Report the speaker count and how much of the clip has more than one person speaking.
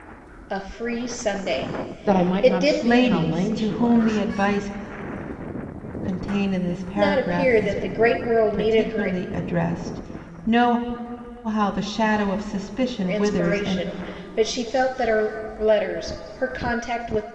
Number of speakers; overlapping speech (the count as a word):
three, about 26%